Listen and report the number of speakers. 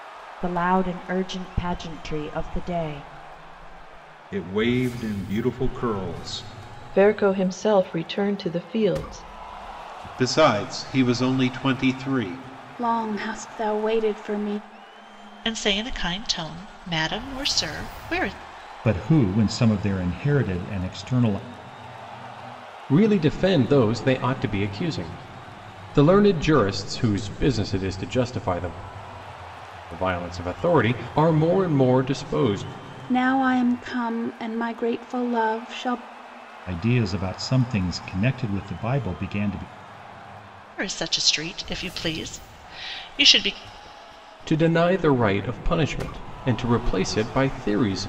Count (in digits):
8